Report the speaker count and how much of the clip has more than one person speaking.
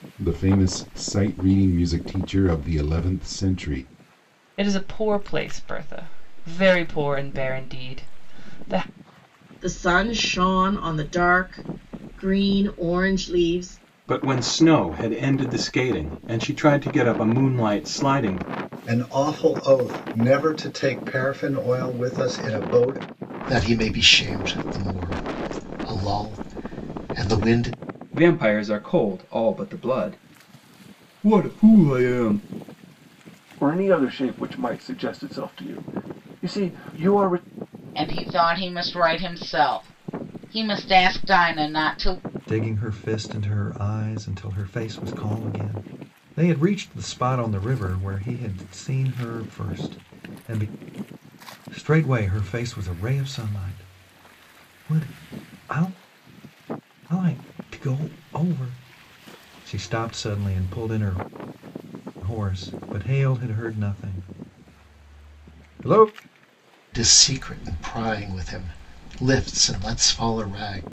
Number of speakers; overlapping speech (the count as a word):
ten, no overlap